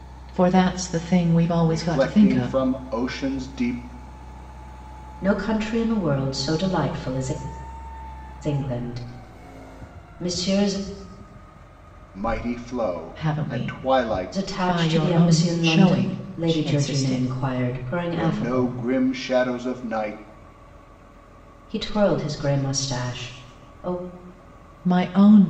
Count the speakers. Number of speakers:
3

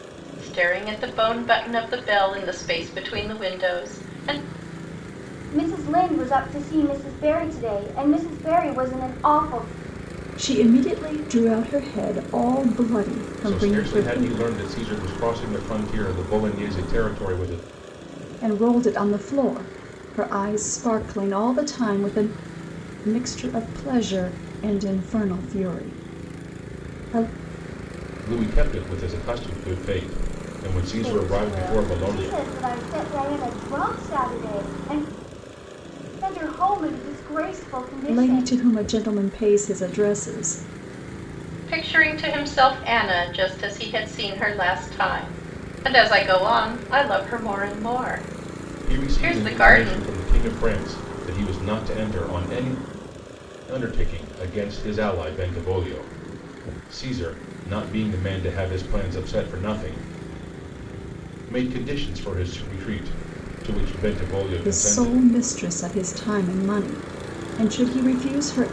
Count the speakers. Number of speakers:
4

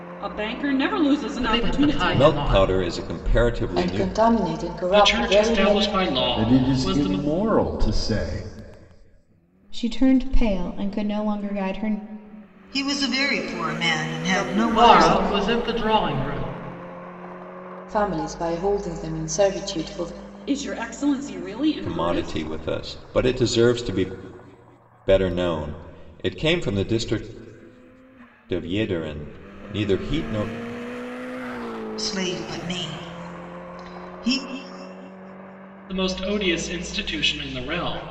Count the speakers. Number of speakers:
8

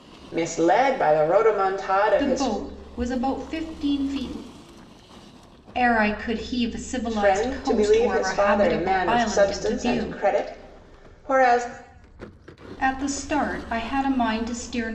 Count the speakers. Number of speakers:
2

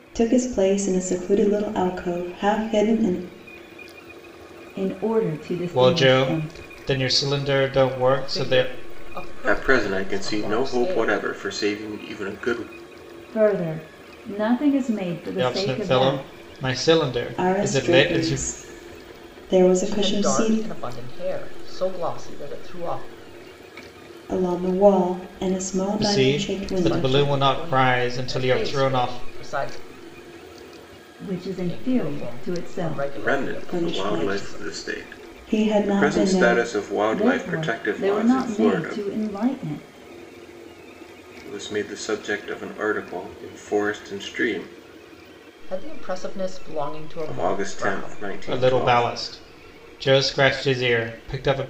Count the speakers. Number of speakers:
5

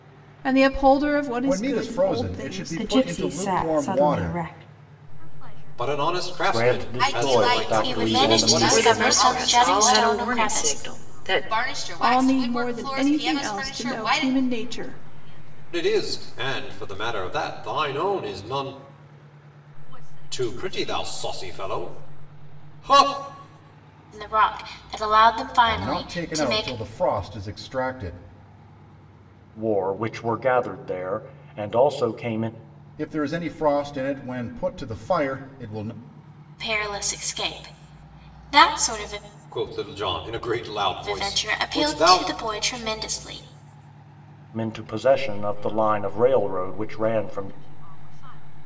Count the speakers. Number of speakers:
9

